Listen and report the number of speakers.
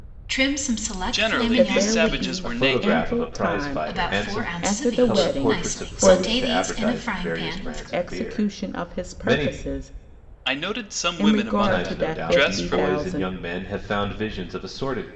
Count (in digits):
4